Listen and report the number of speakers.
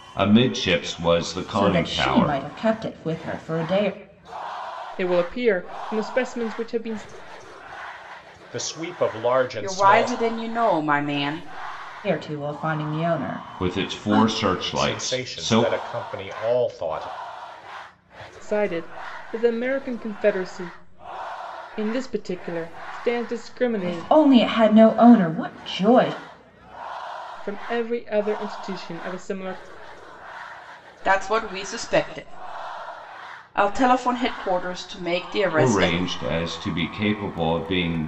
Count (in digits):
5